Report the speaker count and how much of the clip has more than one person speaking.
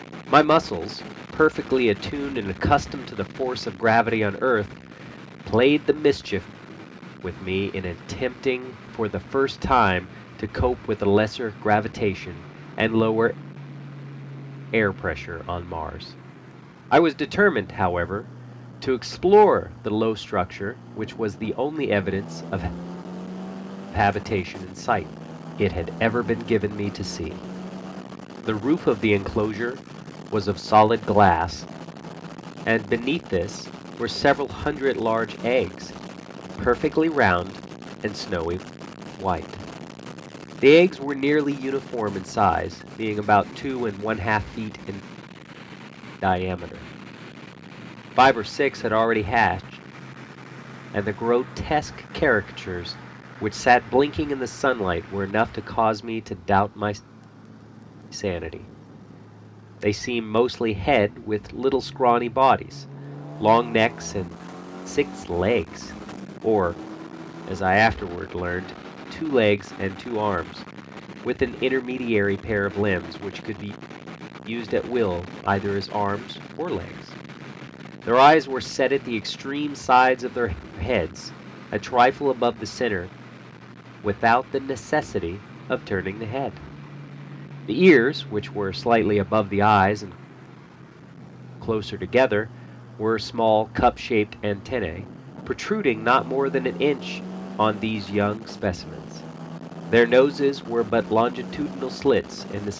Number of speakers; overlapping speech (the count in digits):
1, no overlap